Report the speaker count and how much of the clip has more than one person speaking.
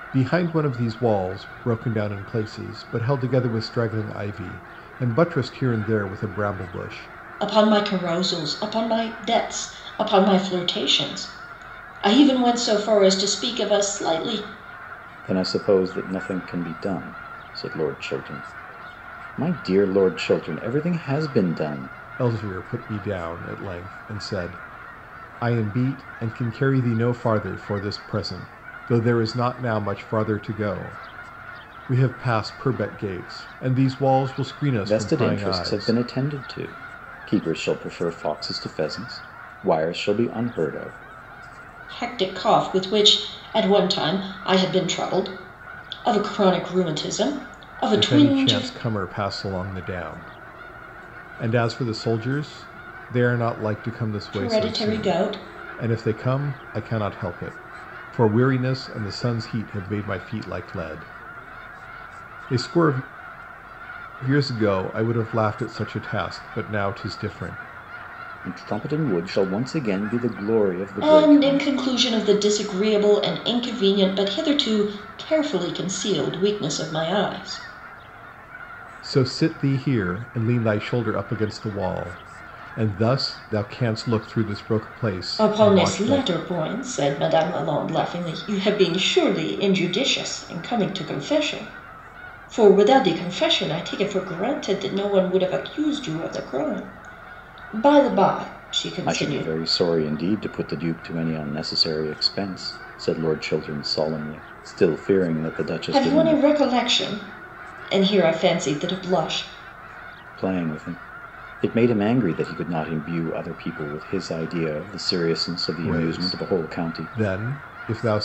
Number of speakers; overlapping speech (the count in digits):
3, about 6%